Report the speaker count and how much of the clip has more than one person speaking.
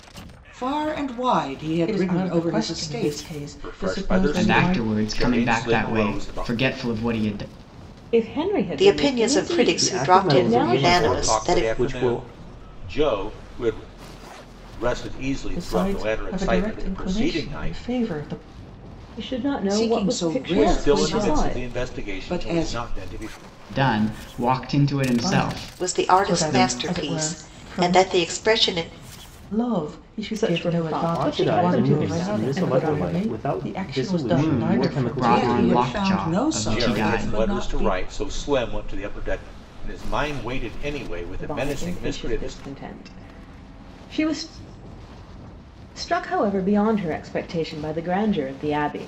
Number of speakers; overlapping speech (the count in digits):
7, about 51%